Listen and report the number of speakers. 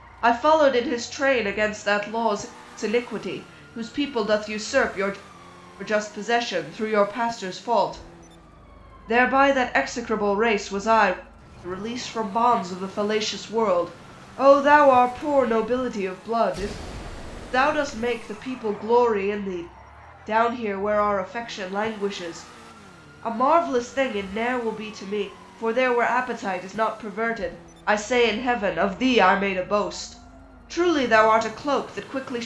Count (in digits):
1